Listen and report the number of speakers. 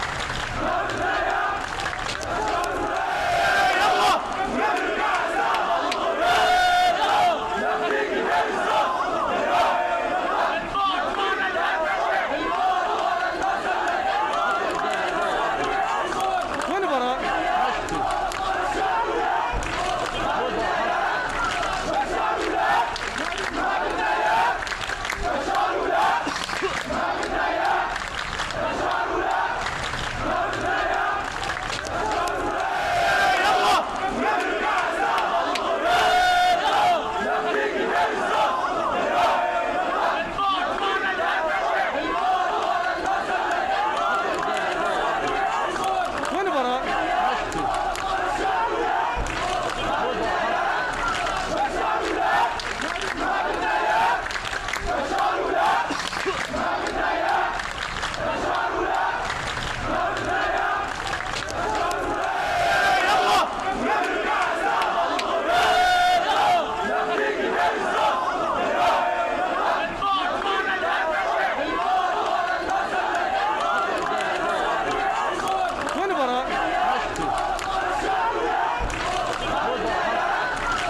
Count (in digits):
0